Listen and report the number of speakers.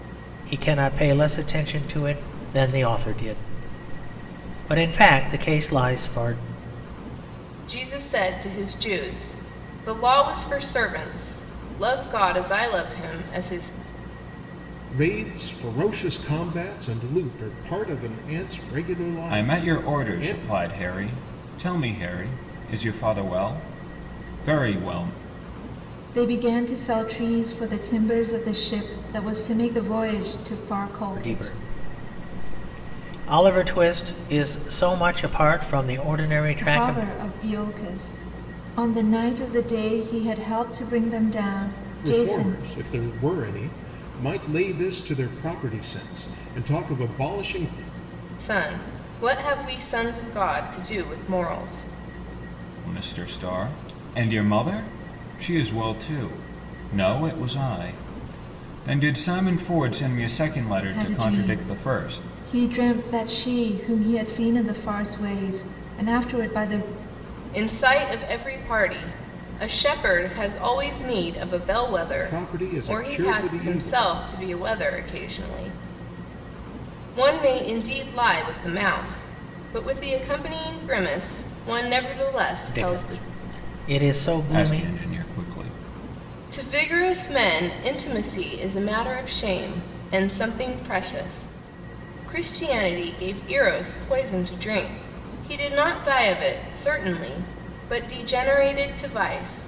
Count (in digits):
5